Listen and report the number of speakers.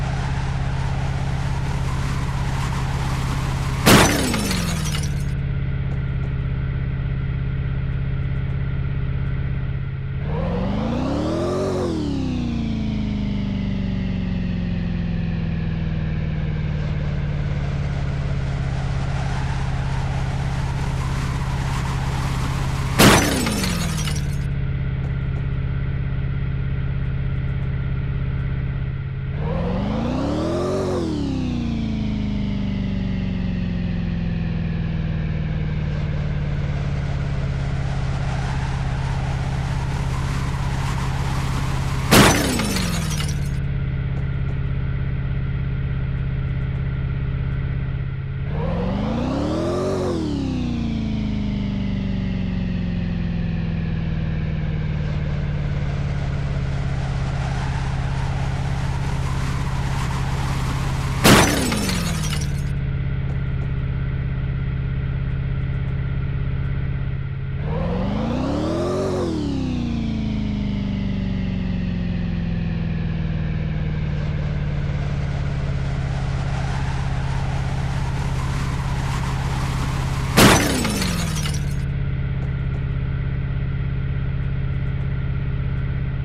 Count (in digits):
0